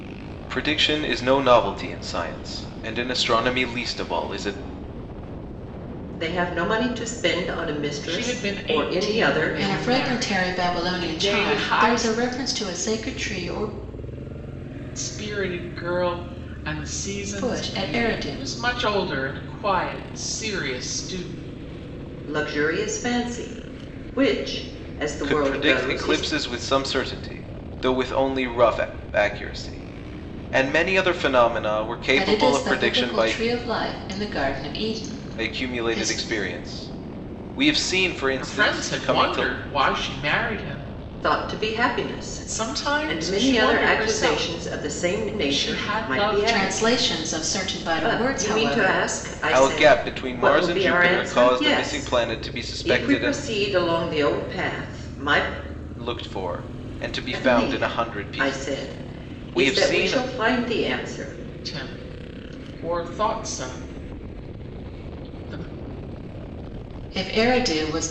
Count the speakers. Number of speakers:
four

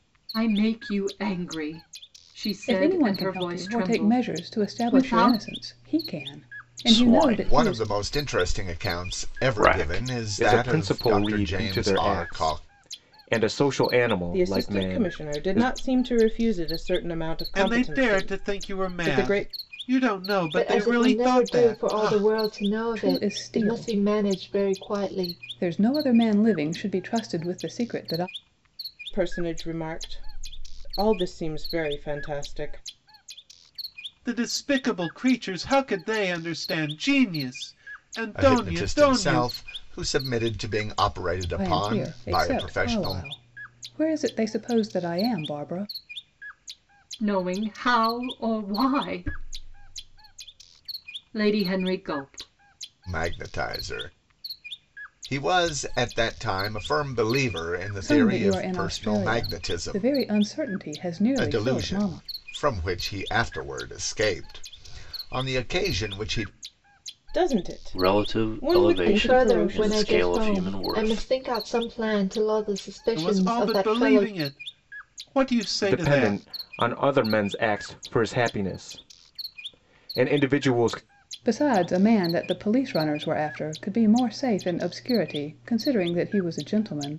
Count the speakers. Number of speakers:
eight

